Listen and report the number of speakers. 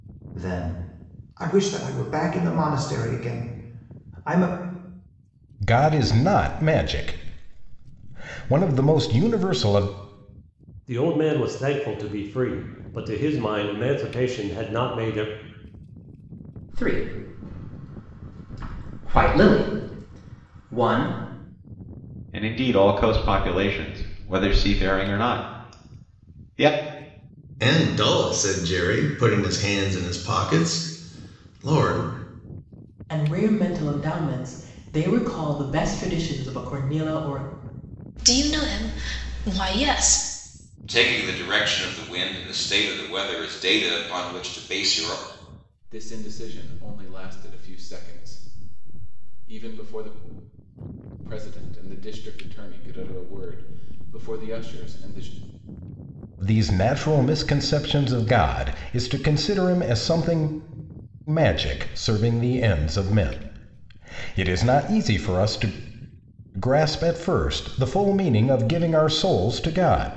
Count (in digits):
10